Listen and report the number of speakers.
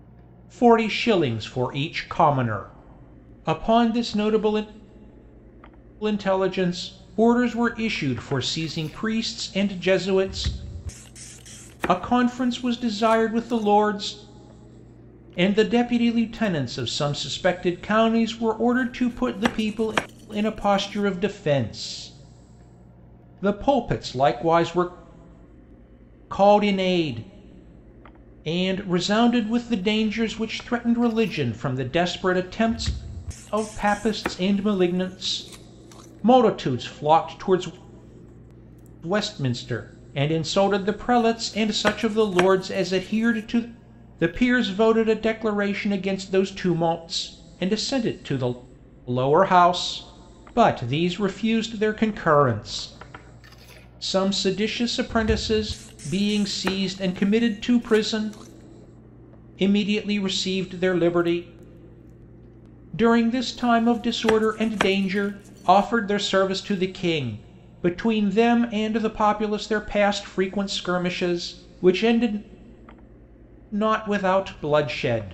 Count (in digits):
1